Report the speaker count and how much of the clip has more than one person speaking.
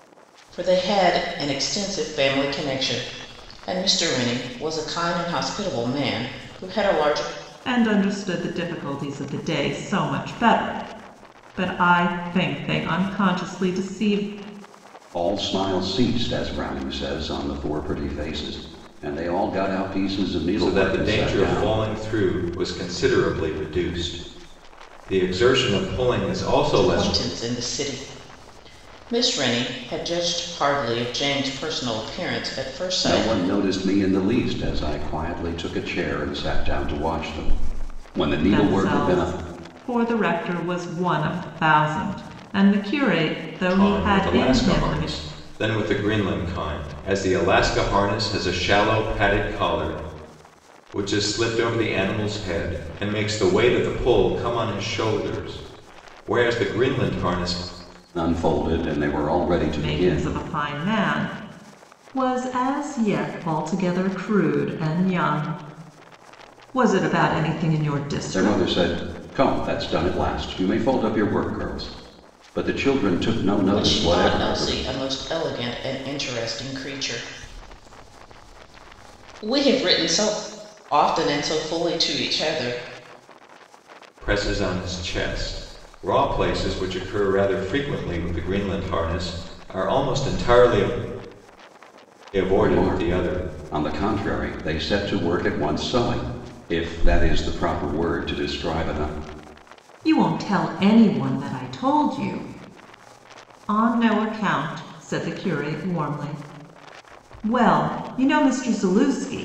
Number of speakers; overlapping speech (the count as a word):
four, about 7%